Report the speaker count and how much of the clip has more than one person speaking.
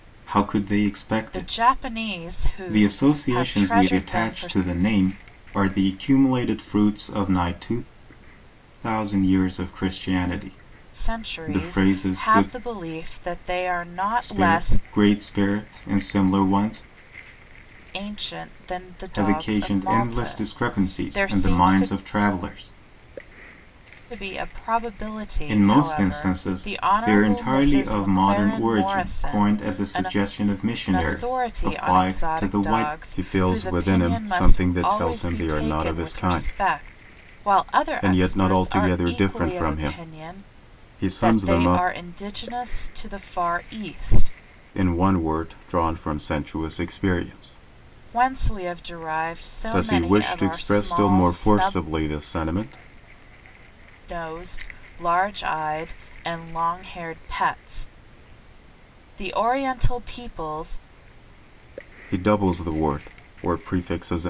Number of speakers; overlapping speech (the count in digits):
2, about 37%